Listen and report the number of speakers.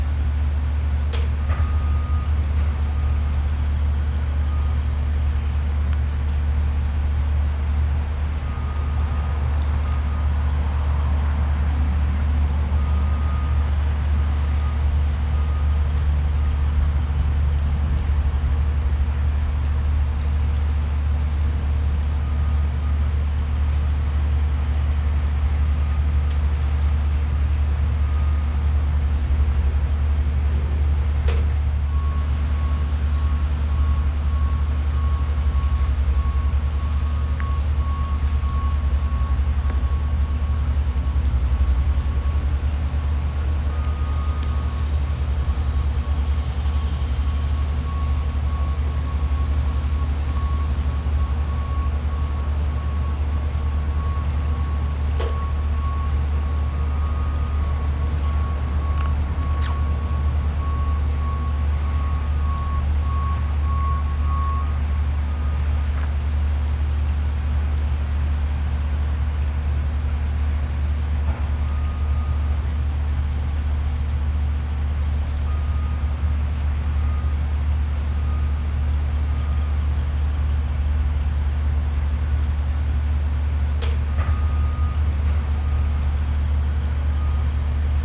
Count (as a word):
zero